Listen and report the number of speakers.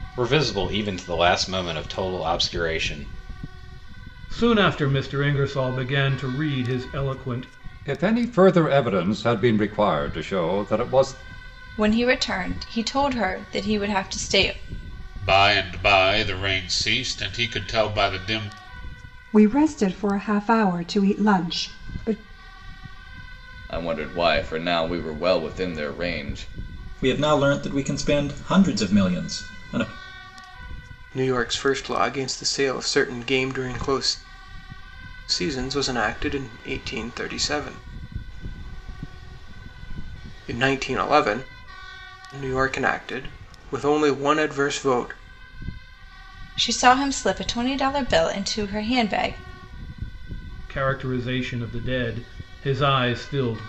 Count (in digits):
9